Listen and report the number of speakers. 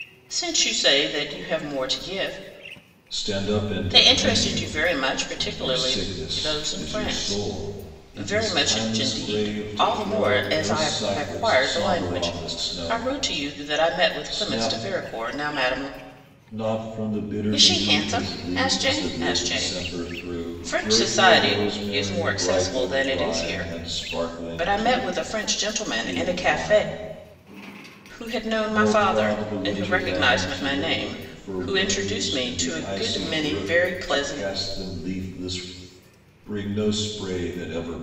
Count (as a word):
two